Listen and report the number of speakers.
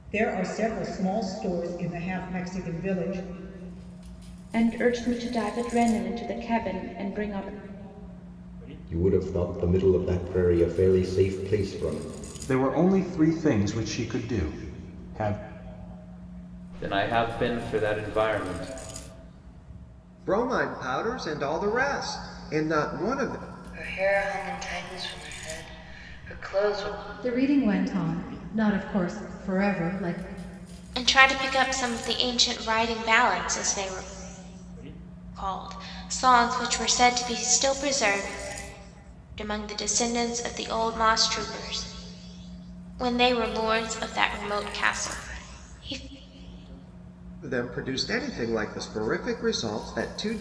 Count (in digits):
9